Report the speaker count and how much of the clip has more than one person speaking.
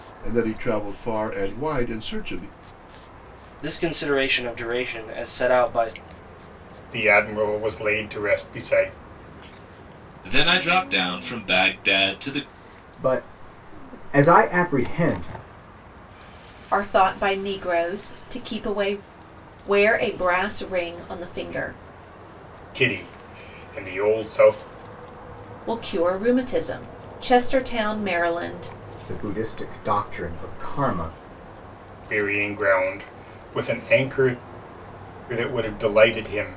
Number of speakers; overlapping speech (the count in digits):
6, no overlap